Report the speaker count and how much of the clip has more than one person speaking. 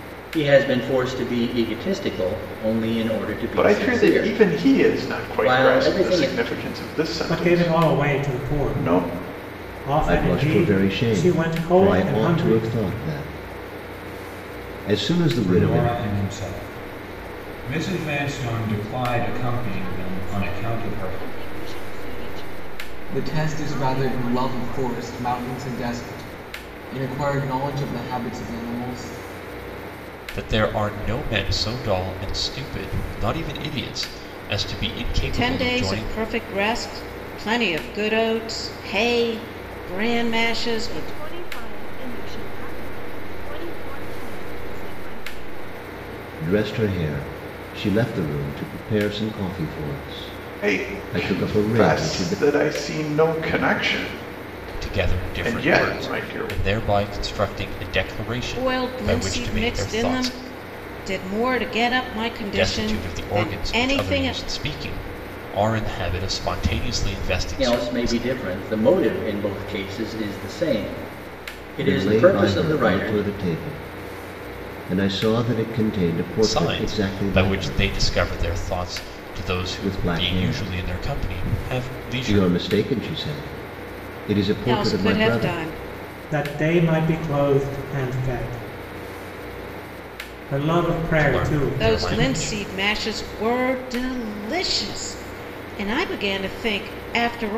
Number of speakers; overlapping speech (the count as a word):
nine, about 31%